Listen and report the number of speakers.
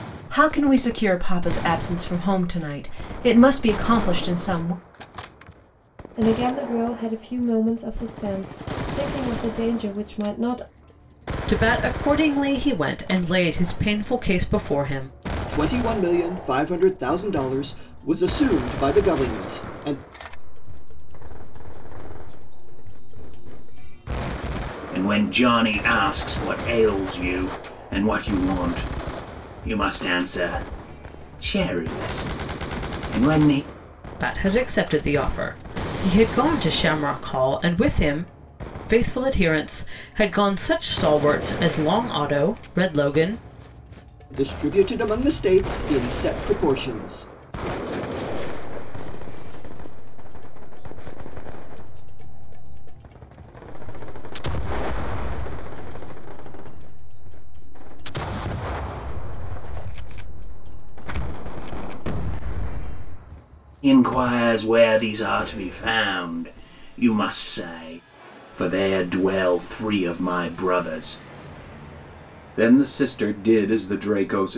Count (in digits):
6